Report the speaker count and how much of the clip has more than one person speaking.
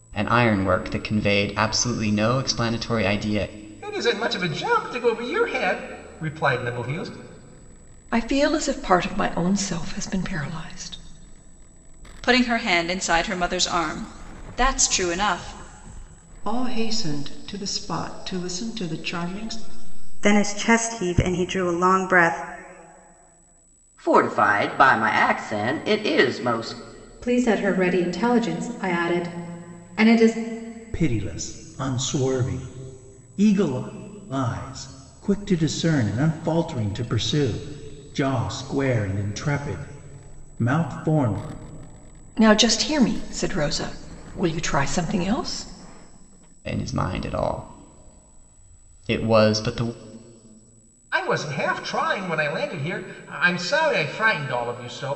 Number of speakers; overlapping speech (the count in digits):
9, no overlap